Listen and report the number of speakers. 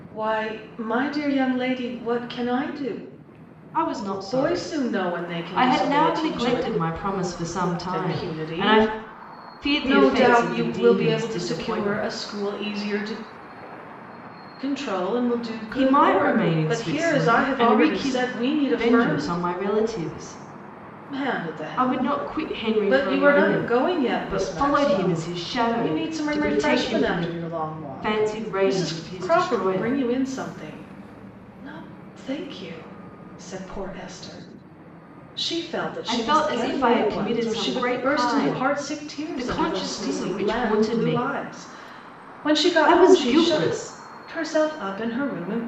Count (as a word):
two